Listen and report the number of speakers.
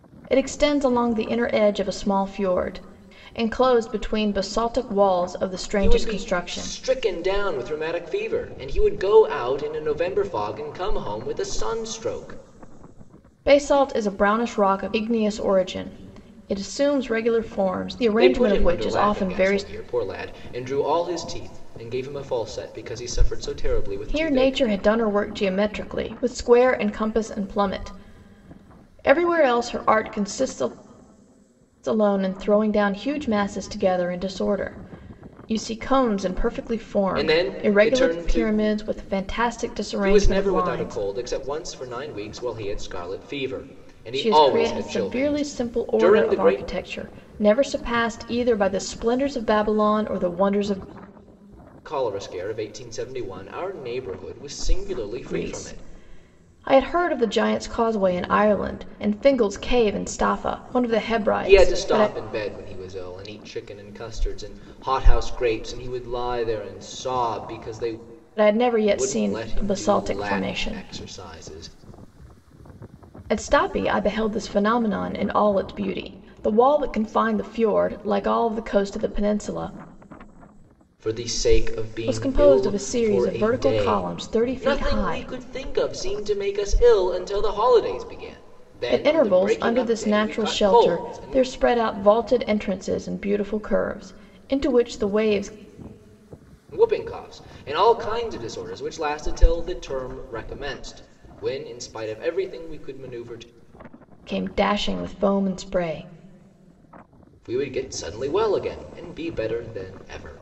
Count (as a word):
two